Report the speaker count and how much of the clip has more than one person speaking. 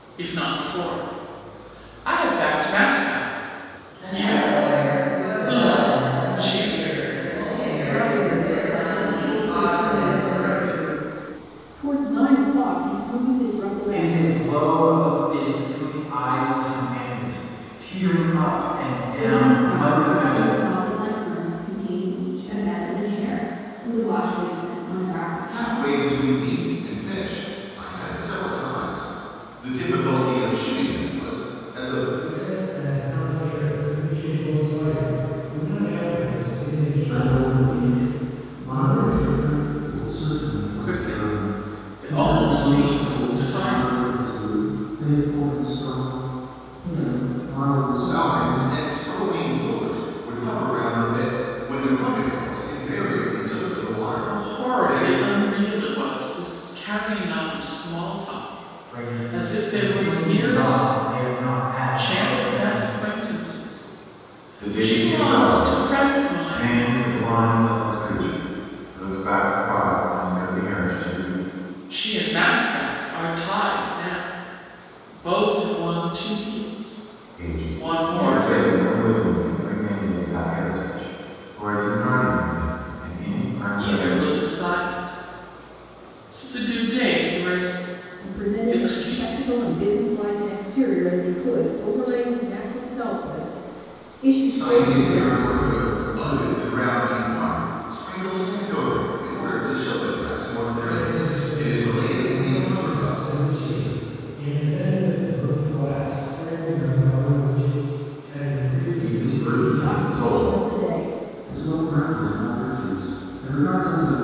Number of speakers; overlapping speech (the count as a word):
eight, about 26%